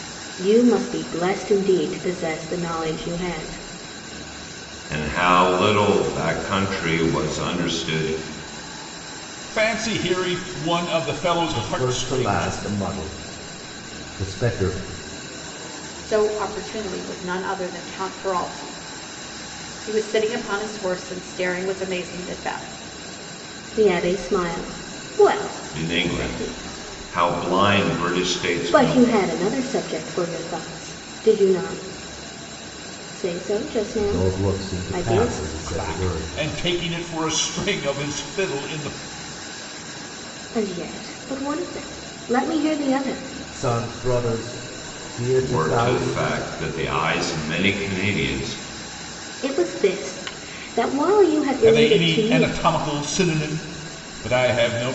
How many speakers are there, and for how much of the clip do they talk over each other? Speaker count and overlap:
5, about 12%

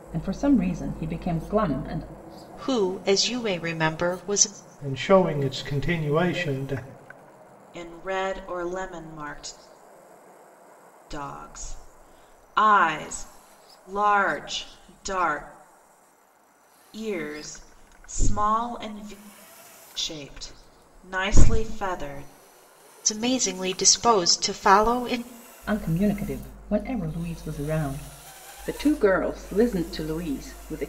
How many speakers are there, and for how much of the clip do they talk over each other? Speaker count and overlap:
4, no overlap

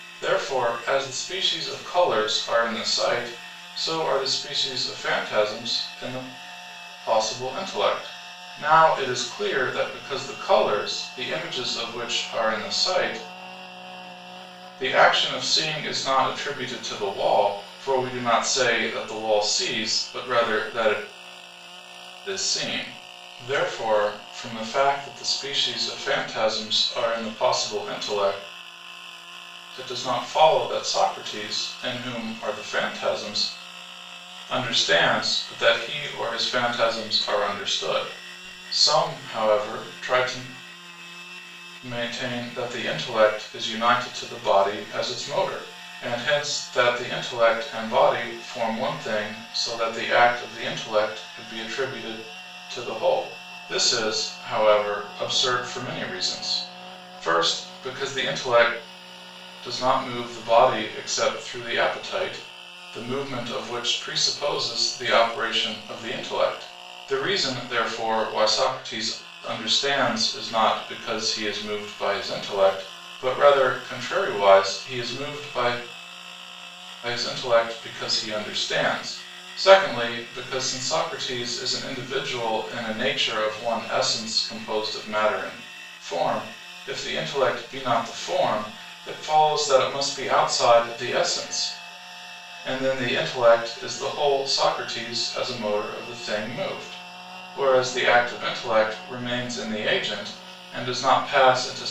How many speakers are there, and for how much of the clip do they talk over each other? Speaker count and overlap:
1, no overlap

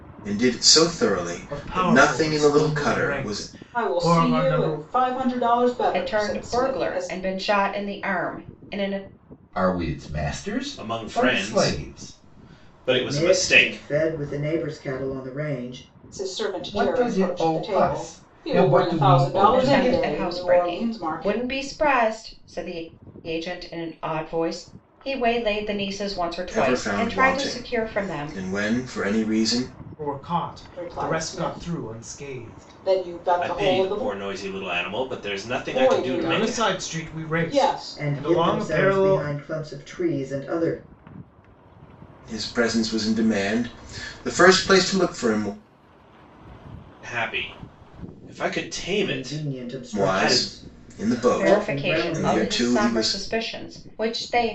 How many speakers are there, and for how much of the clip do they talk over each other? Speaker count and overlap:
7, about 44%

